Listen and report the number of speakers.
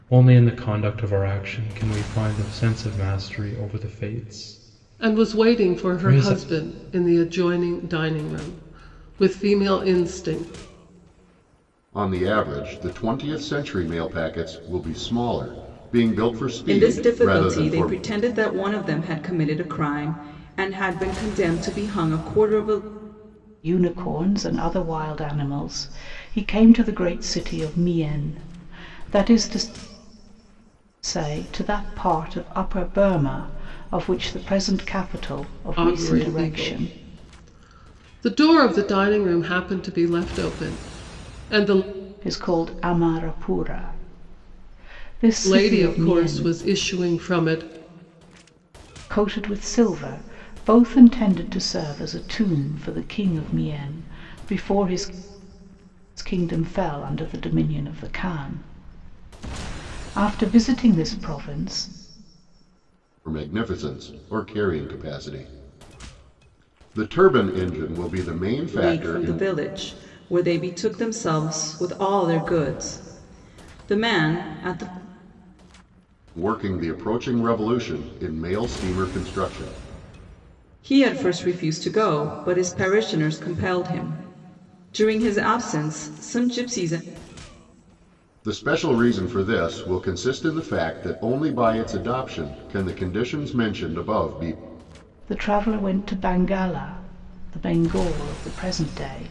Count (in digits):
5